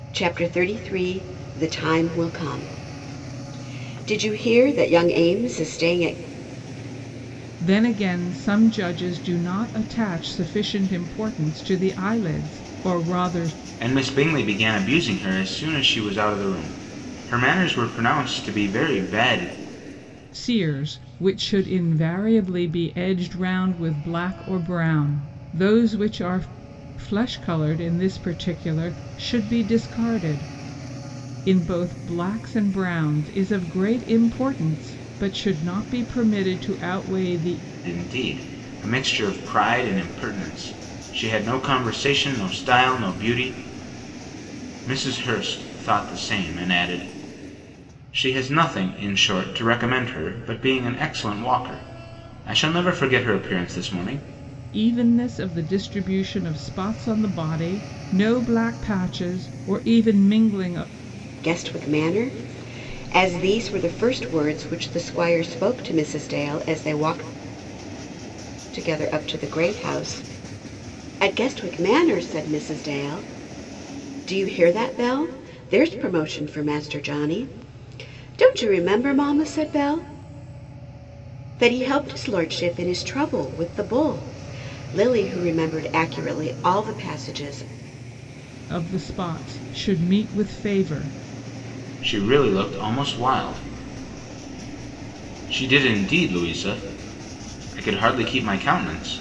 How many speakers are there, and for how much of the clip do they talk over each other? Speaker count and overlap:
three, no overlap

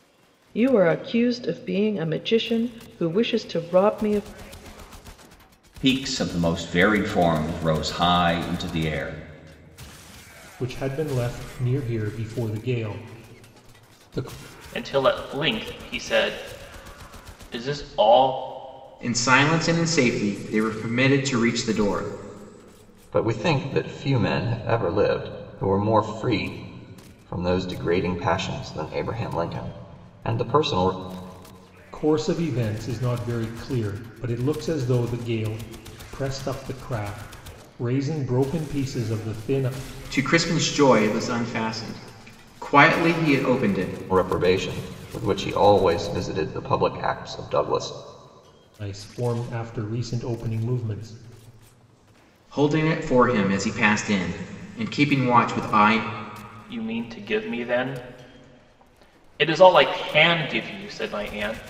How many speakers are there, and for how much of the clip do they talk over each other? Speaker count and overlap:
six, no overlap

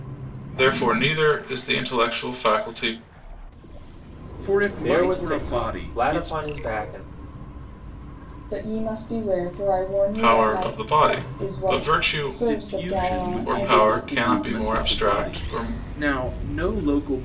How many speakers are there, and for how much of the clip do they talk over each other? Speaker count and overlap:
four, about 39%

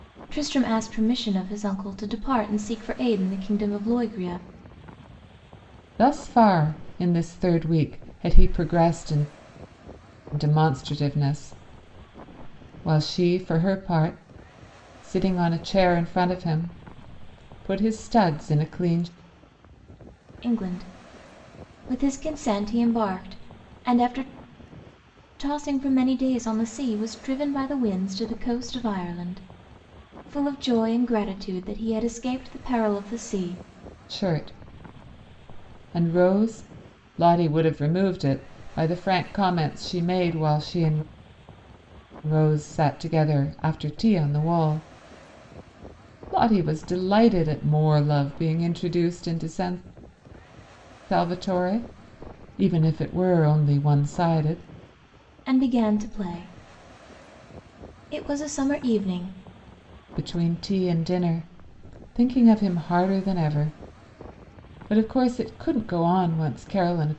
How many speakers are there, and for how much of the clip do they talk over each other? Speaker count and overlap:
two, no overlap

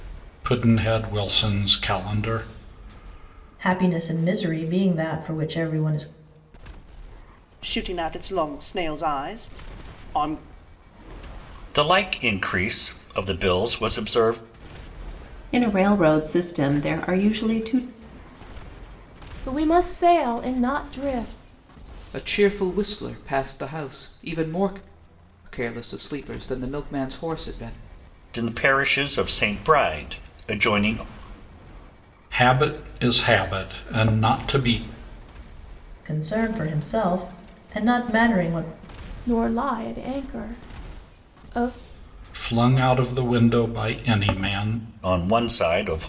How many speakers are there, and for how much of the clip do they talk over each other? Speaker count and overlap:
seven, no overlap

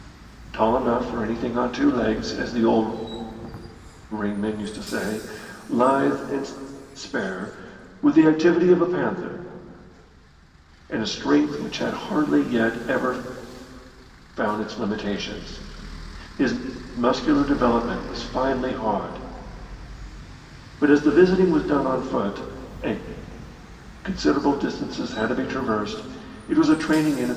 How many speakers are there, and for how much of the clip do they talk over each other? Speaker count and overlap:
one, no overlap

